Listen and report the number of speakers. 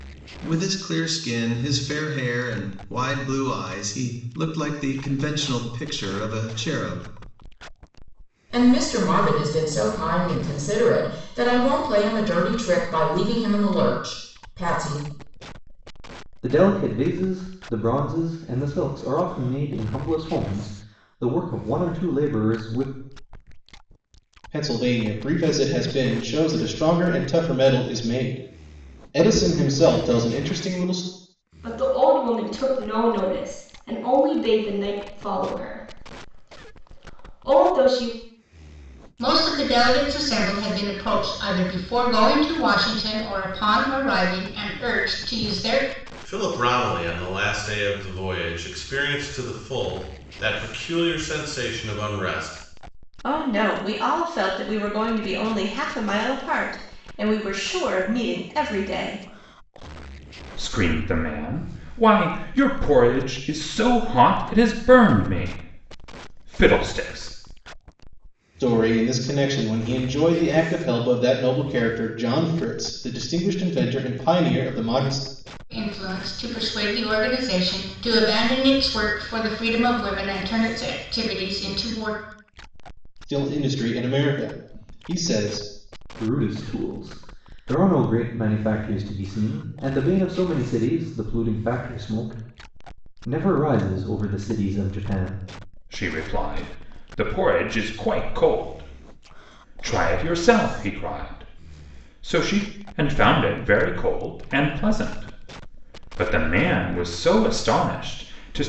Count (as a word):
nine